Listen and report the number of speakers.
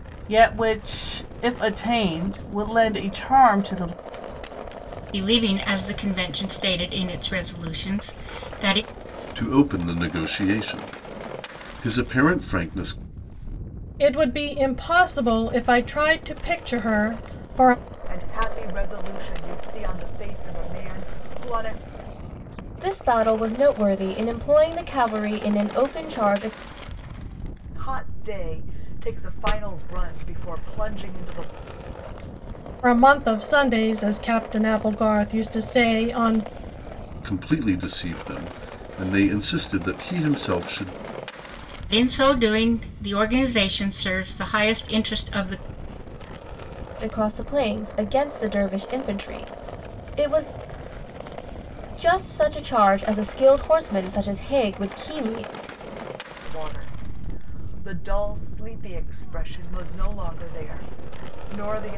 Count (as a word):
six